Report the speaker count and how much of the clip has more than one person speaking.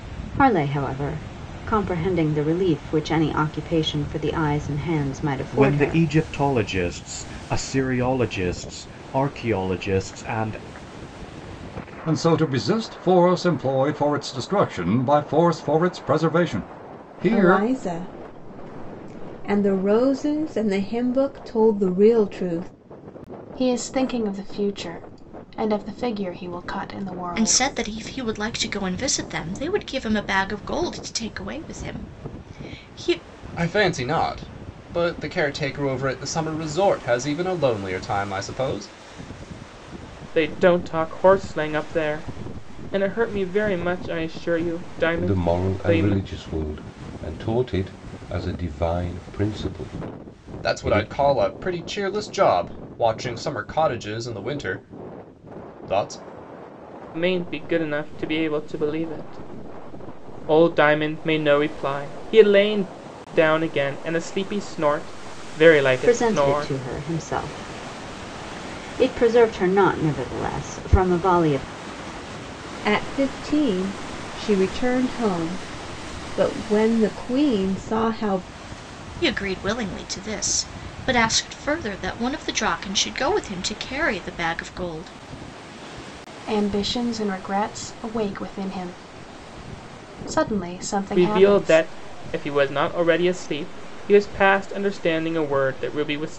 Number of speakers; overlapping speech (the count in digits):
9, about 4%